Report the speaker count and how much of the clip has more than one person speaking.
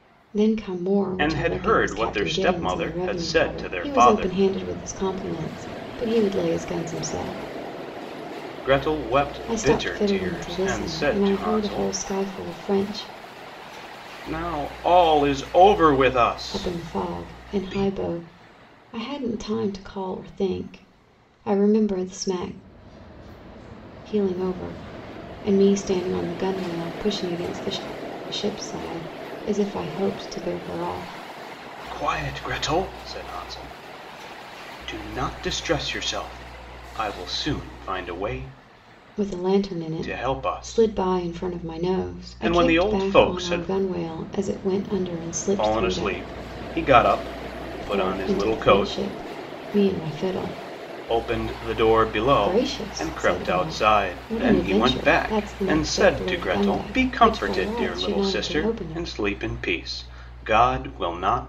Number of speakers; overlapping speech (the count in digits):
2, about 32%